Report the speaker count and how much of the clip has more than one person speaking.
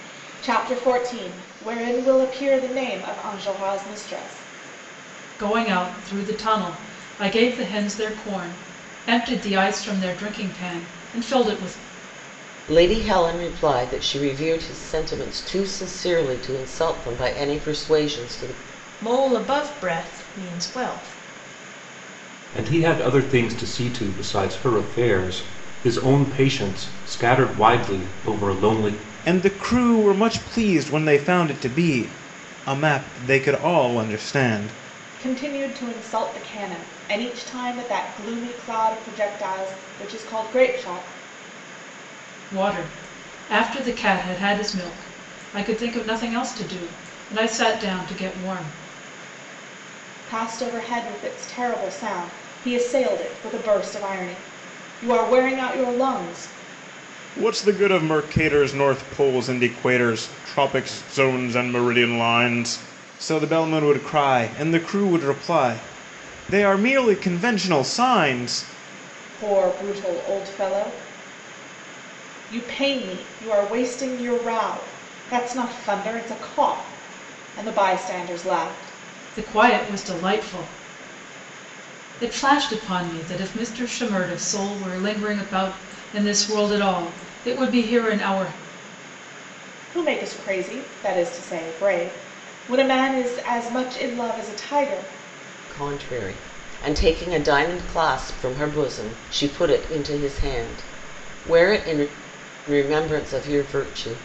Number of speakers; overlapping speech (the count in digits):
6, no overlap